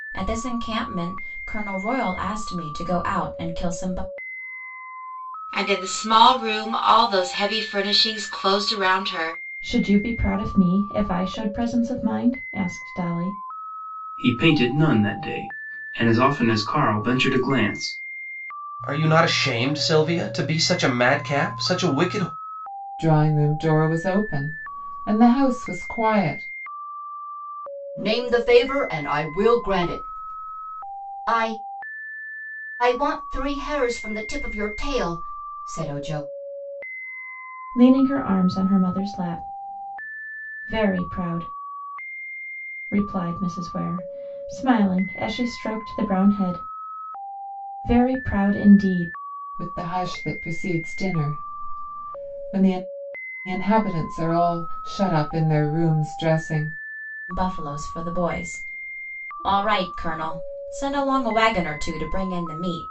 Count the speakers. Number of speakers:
seven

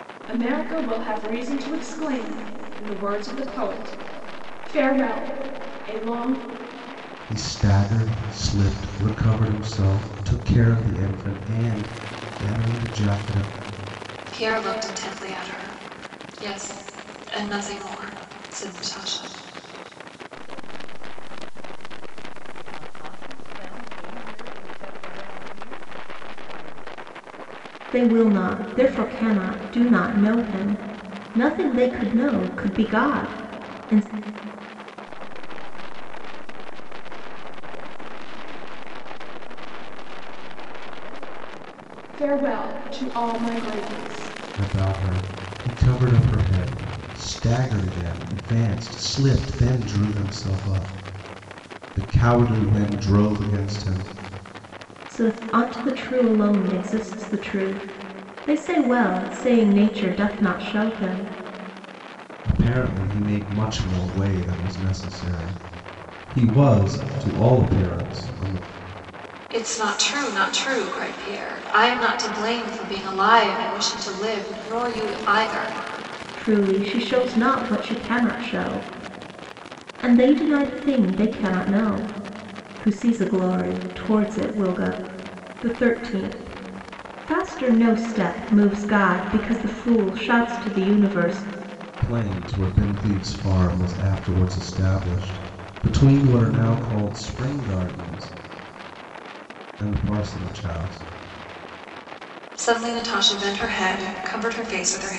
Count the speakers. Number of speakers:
five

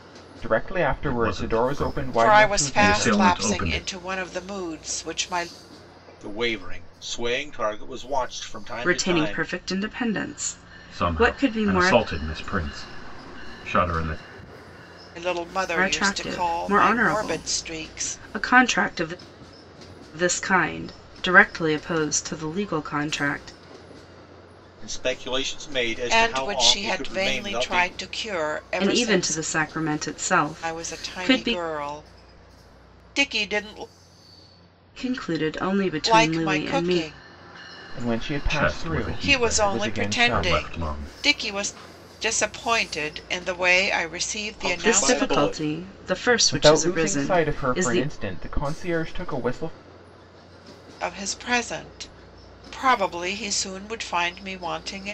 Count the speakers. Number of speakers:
five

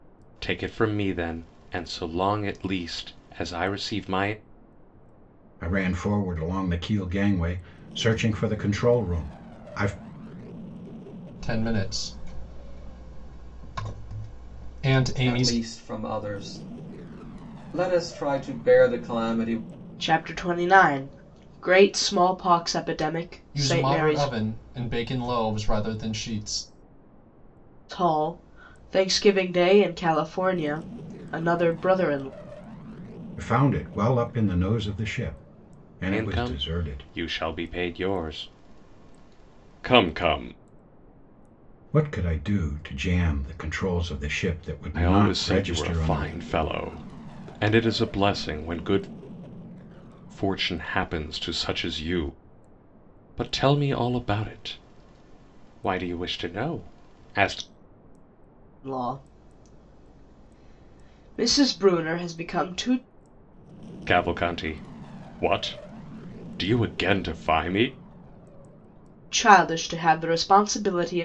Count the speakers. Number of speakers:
five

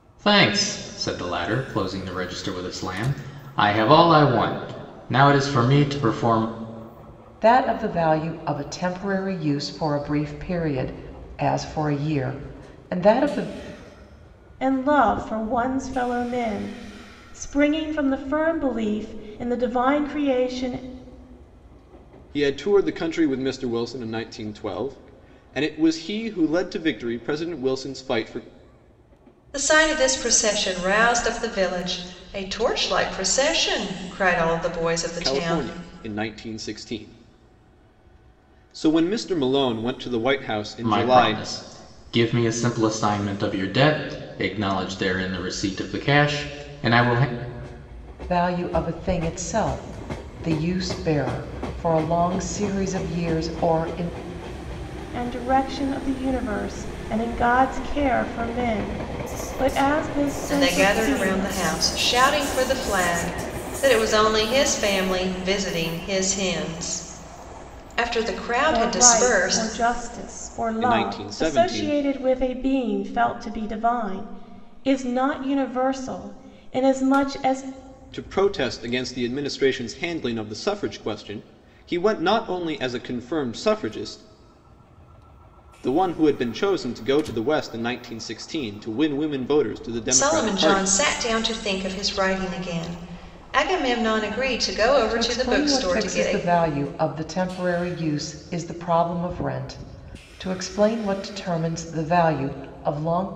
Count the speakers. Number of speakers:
five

